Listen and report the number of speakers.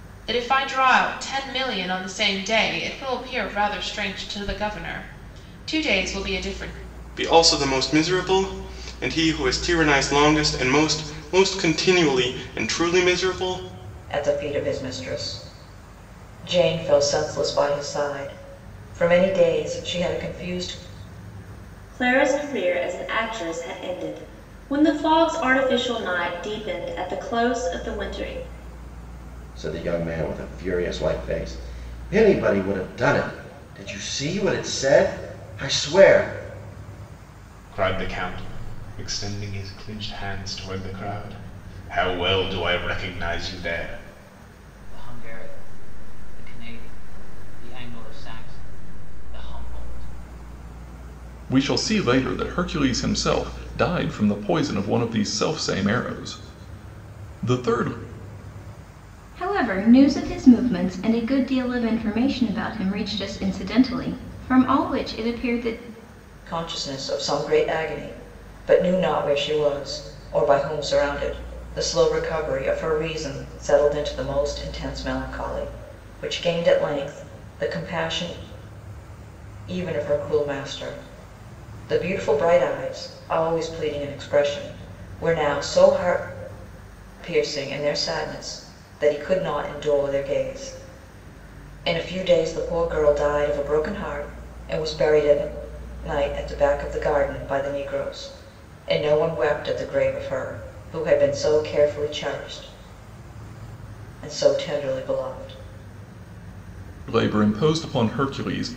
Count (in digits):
9